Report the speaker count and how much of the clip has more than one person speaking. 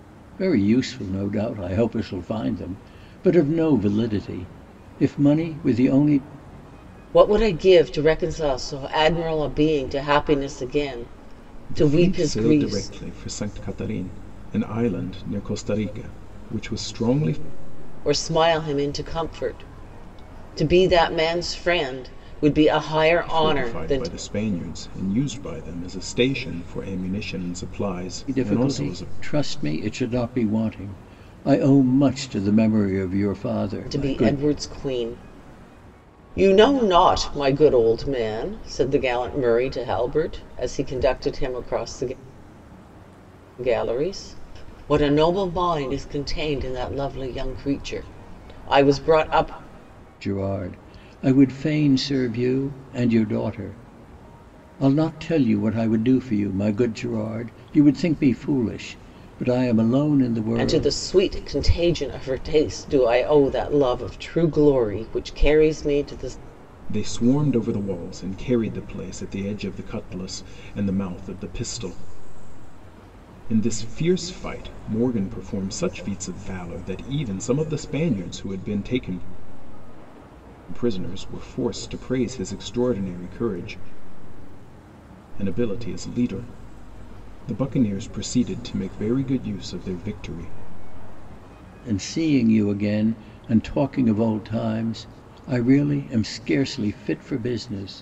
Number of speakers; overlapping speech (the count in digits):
3, about 4%